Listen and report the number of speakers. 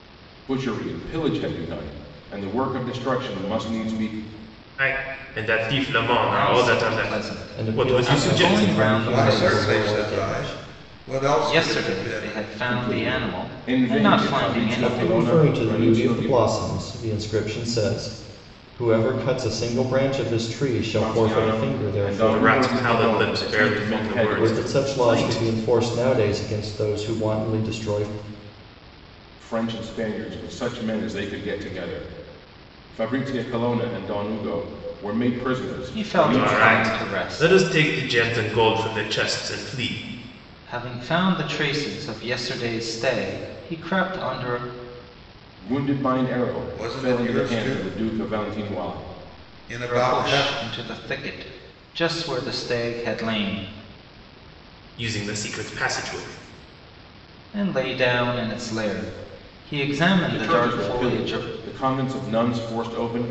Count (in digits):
5